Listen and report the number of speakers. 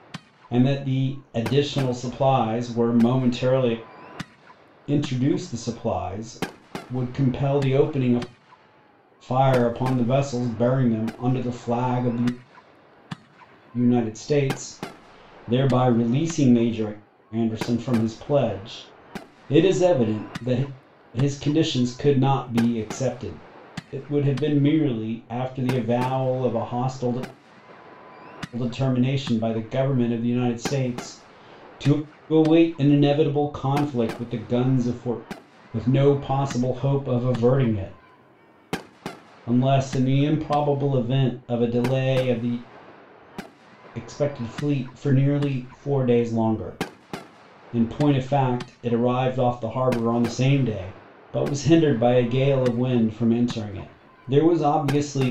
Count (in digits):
1